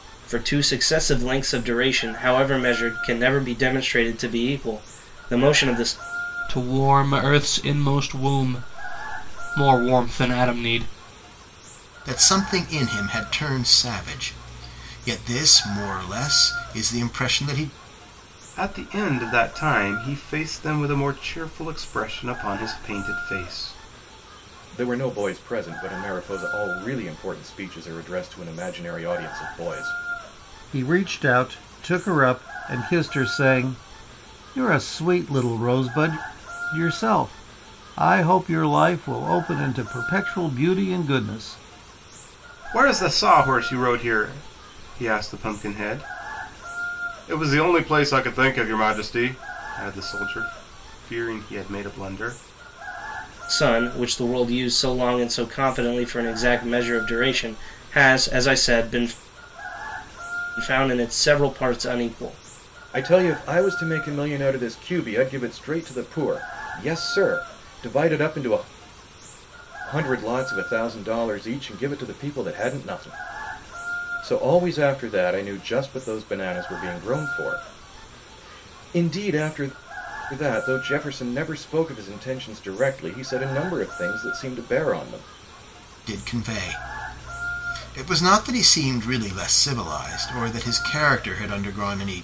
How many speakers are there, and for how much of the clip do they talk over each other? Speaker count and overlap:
6, no overlap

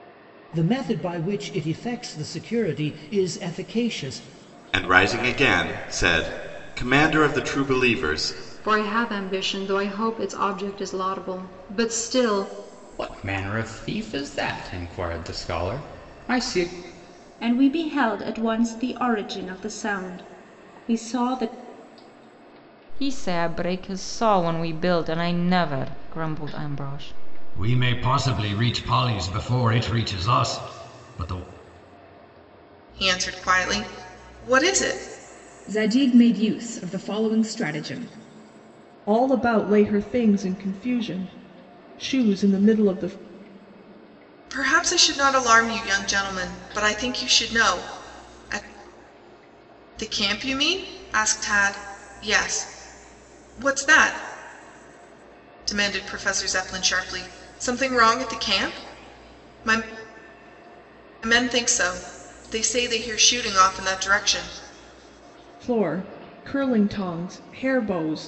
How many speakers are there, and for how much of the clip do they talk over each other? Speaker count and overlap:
10, no overlap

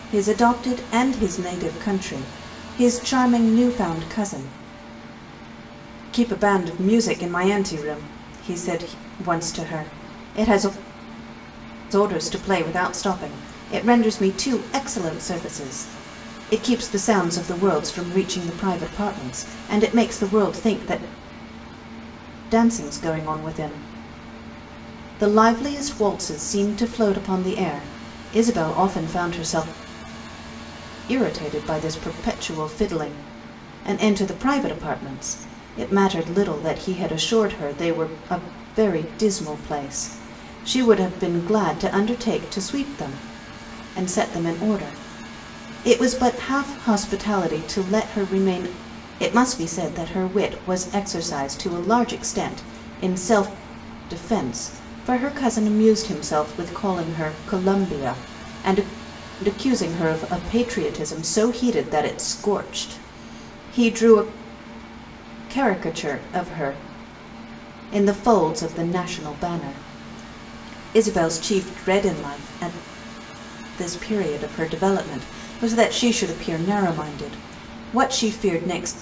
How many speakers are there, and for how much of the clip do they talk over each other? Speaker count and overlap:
1, no overlap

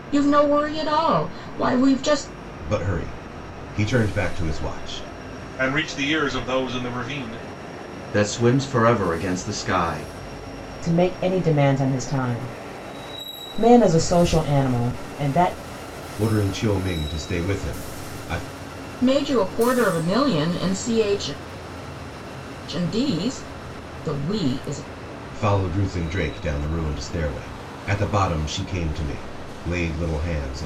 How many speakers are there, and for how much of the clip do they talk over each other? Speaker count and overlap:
5, no overlap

